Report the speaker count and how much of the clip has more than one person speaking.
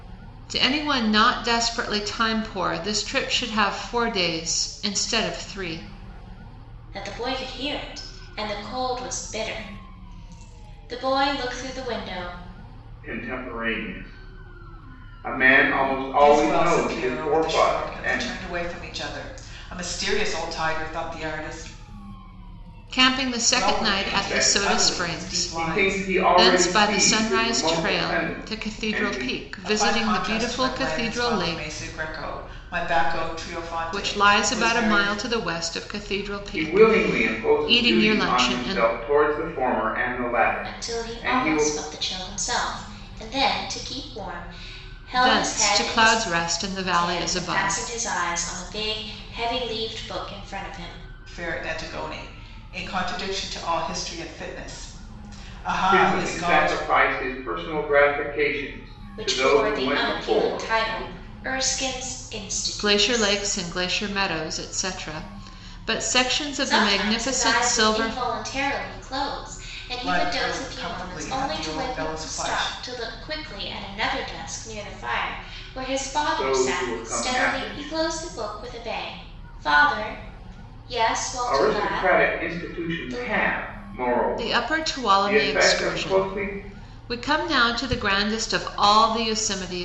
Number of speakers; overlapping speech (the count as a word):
four, about 34%